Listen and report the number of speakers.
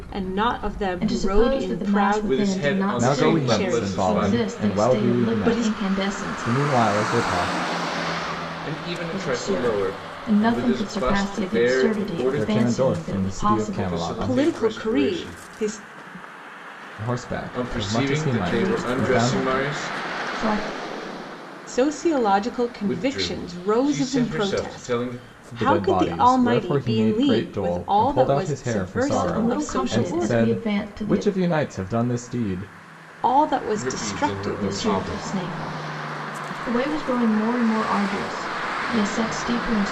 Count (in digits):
4